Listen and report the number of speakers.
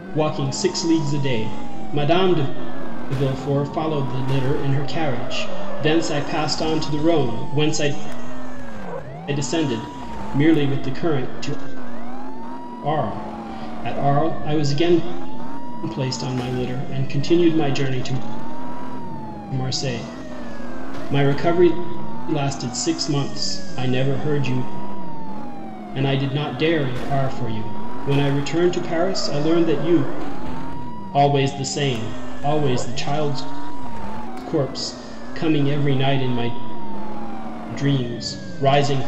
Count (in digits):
1